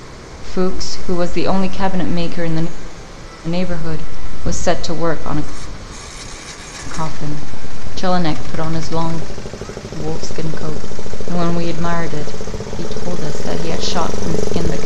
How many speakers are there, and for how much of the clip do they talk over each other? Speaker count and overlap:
1, no overlap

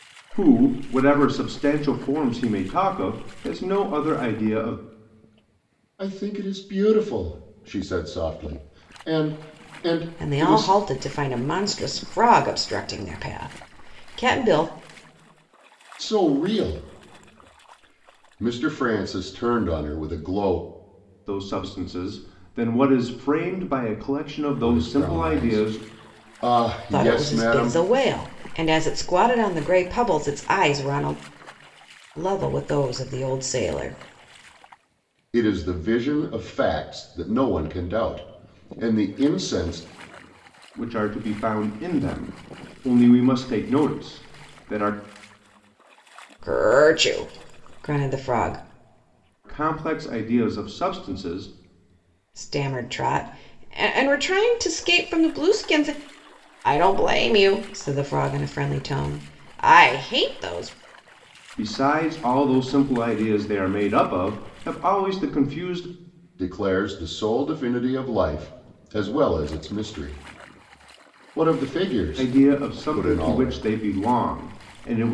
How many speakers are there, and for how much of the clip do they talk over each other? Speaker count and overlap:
3, about 6%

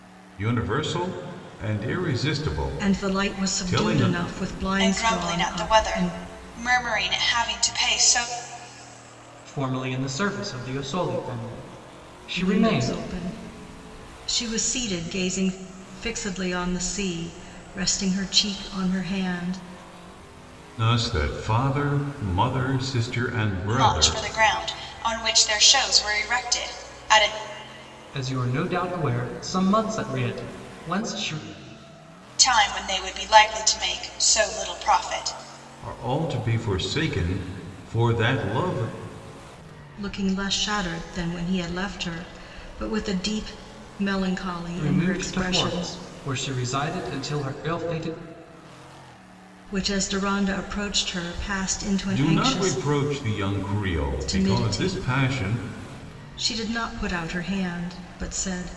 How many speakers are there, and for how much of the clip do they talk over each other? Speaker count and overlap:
4, about 12%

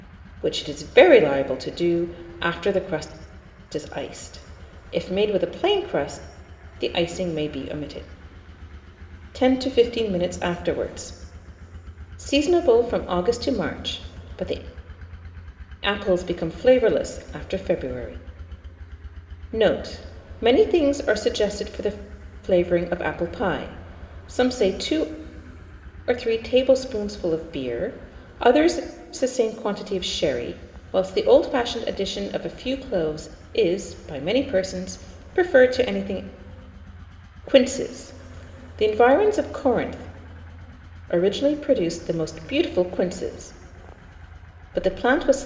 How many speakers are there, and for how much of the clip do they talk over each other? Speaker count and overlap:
1, no overlap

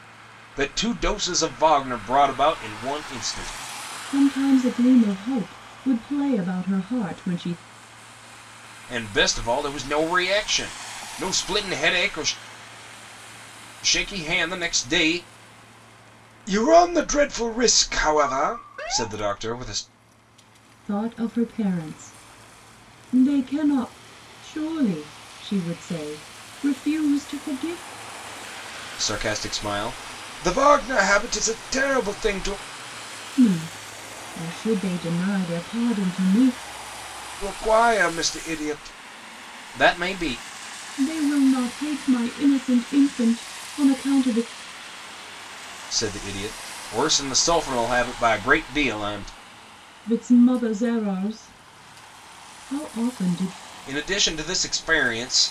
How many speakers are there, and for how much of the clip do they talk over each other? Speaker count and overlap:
2, no overlap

